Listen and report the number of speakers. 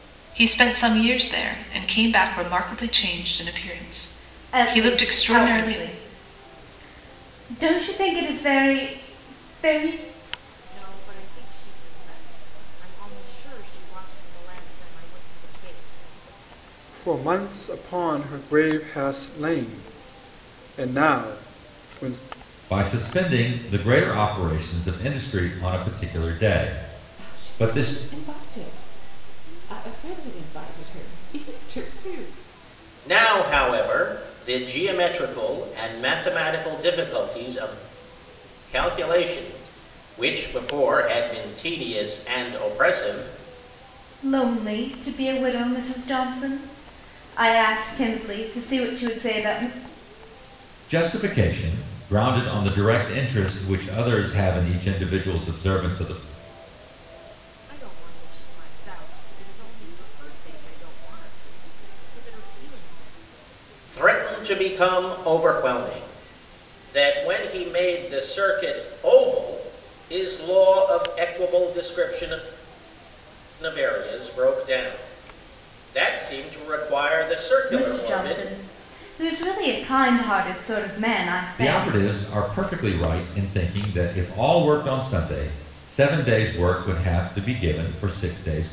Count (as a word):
seven